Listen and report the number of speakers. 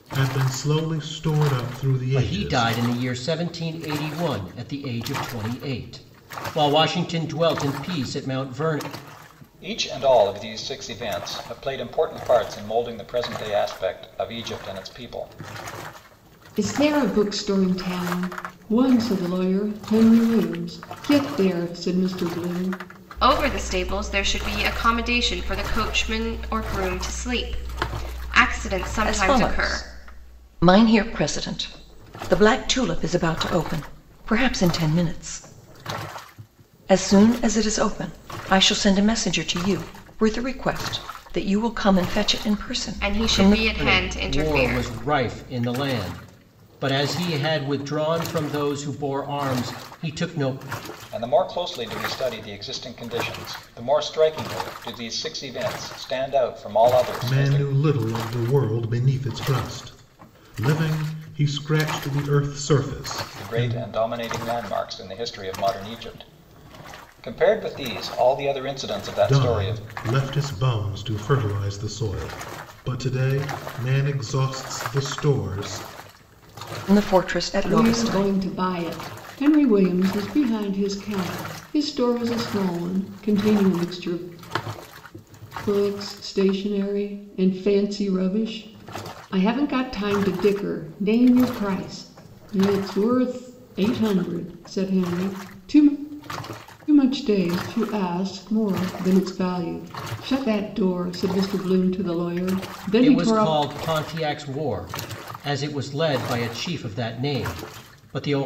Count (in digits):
6